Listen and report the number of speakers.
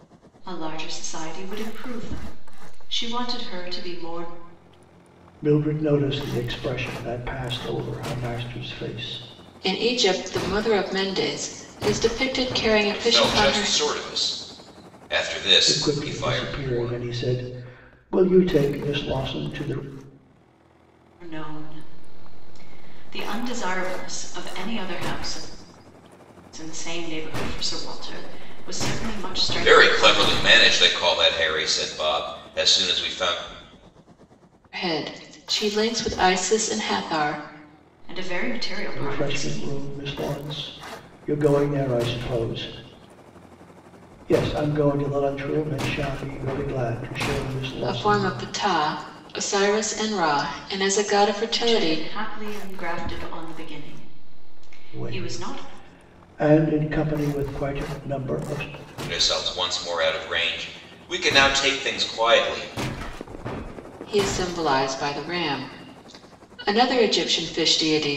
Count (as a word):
four